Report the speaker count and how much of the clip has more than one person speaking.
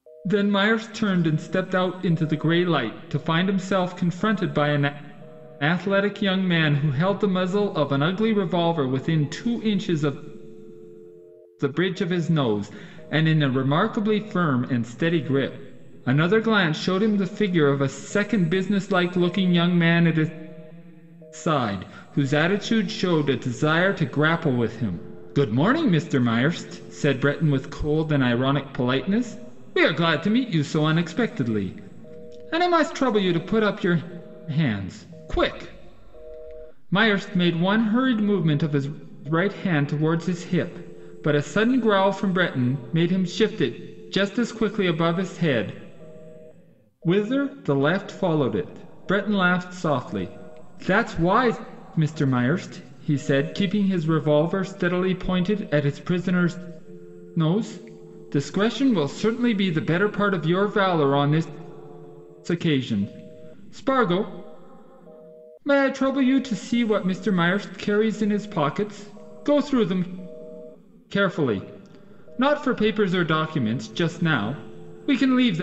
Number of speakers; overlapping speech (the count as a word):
one, no overlap